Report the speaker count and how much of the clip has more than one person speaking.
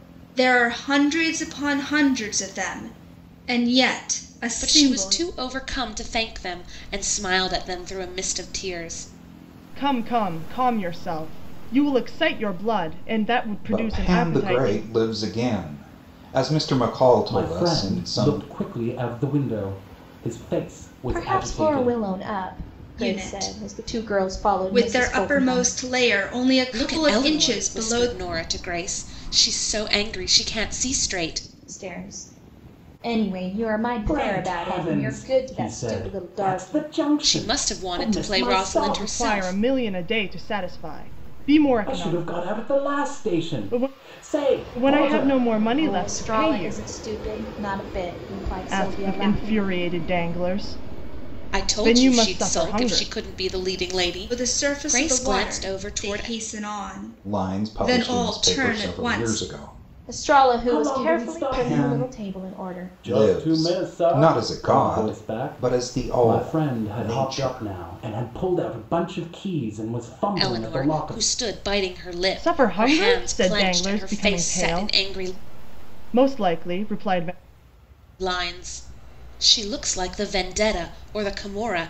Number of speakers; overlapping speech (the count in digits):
6, about 43%